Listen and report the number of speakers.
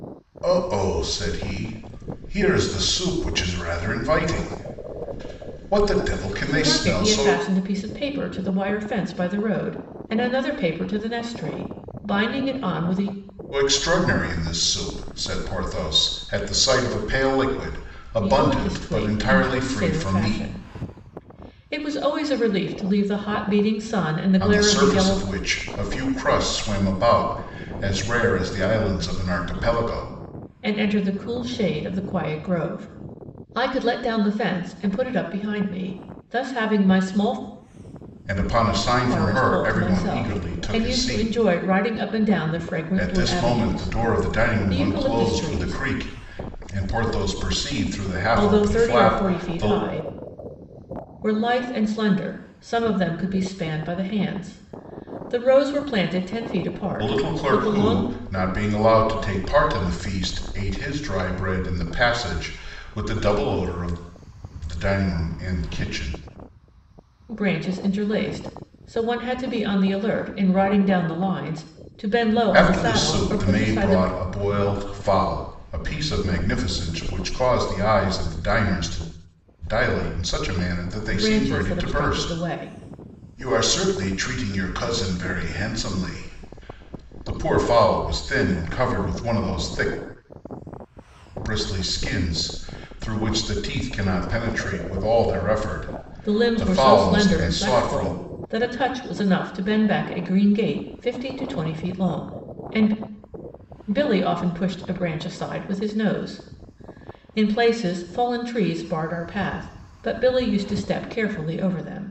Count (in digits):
2